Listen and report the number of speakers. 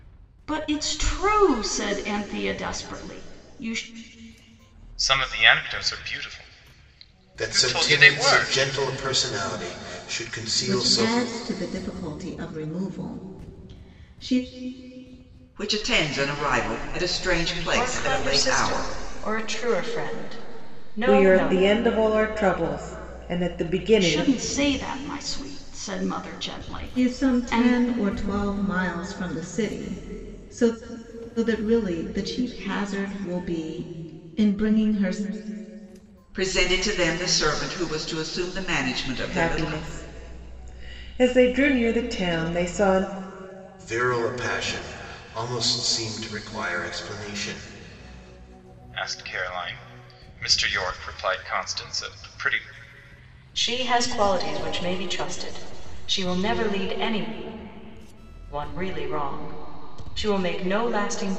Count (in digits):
7